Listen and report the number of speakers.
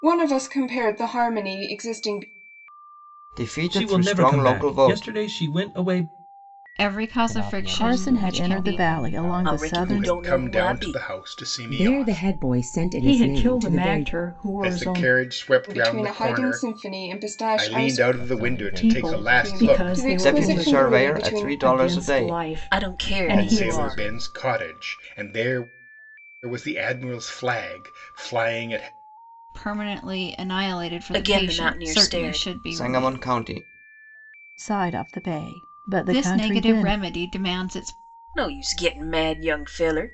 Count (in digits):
10